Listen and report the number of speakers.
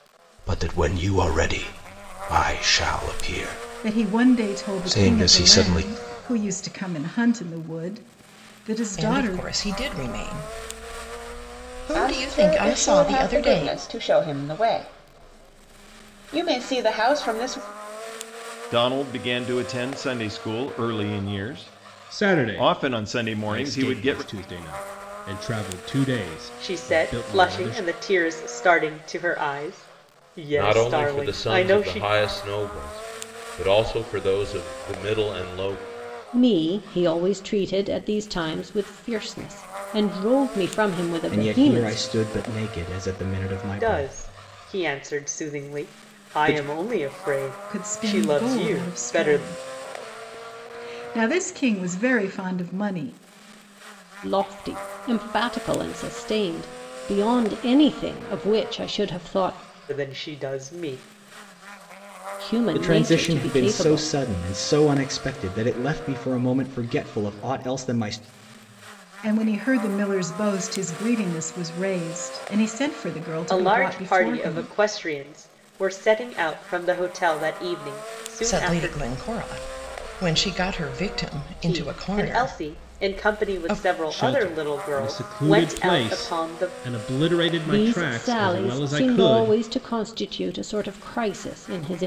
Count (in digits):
10